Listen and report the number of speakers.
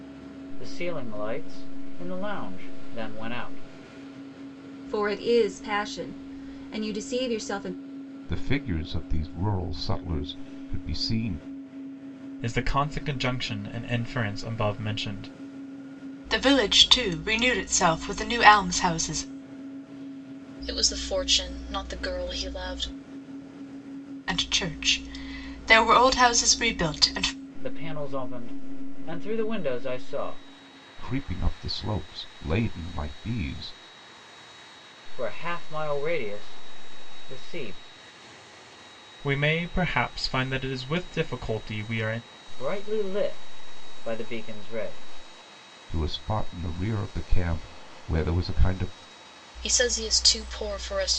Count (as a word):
six